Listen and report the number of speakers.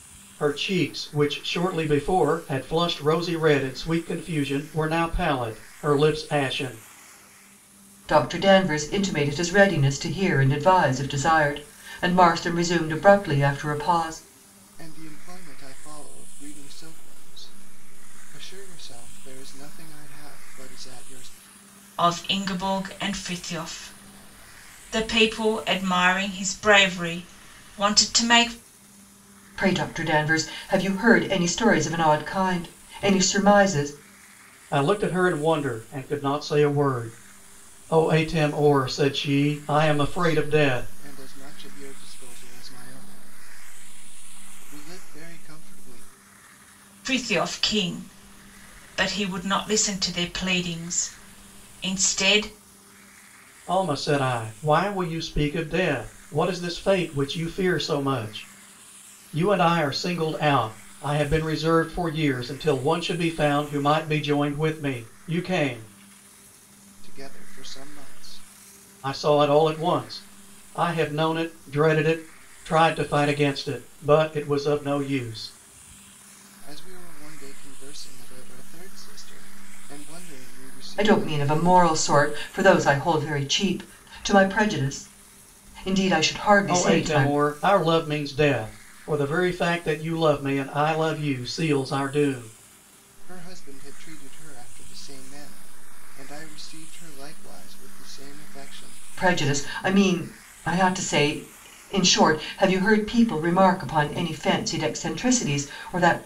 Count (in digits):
4